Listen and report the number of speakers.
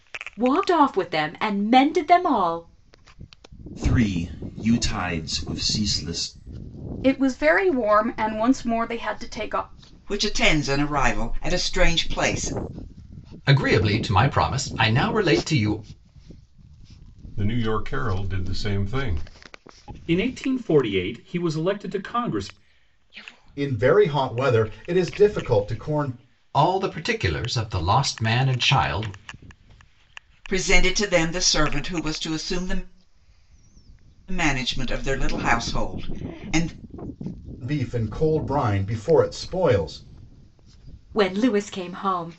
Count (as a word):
eight